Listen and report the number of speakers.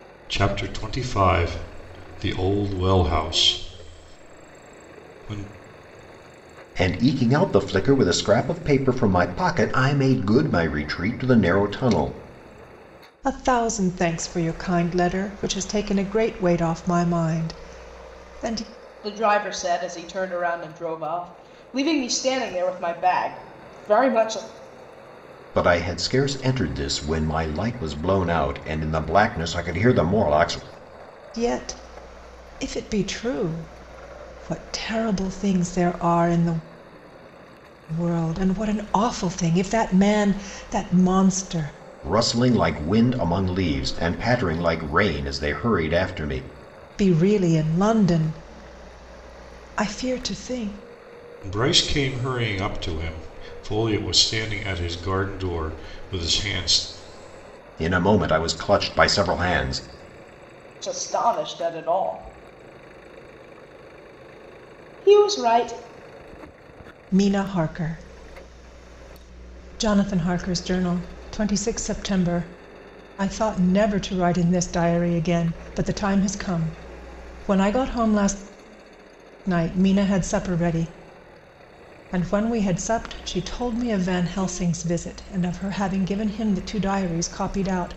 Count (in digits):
4